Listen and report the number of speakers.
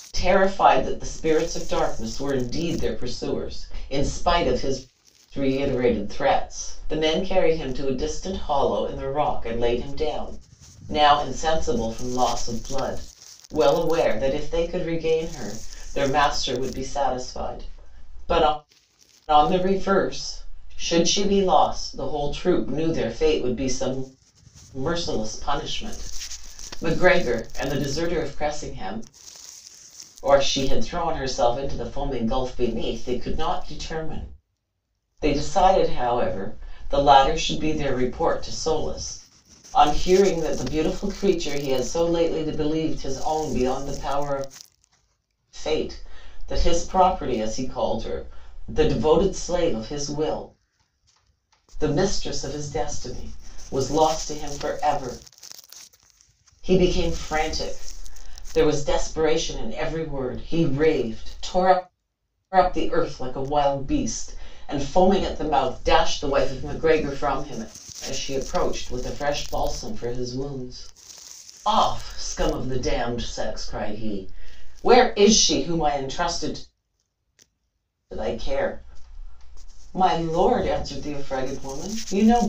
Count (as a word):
one